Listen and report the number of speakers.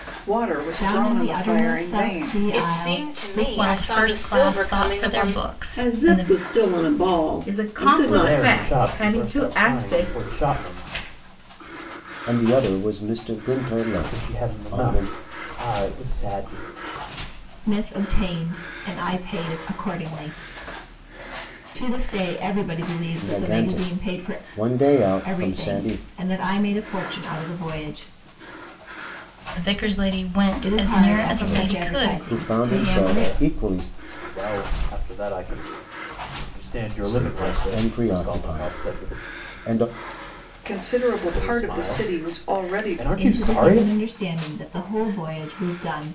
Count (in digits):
8